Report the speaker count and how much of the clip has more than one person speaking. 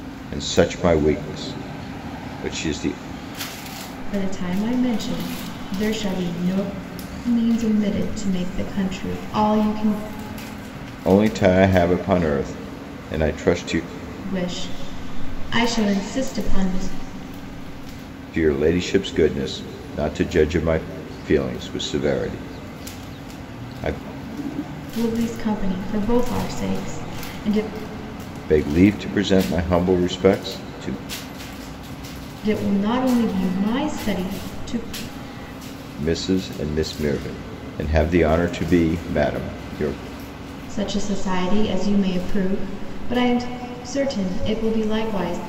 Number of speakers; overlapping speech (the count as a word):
two, no overlap